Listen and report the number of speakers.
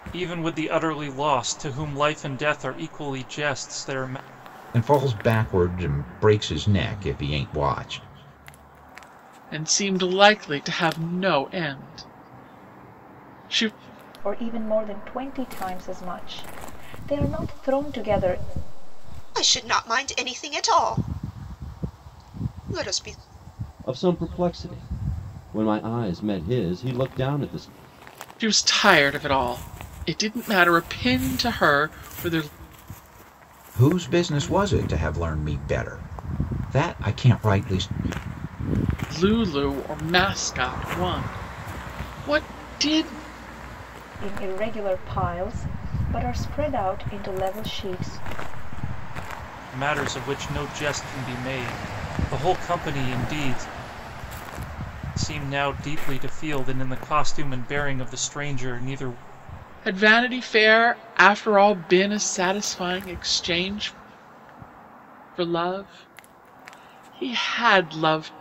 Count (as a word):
six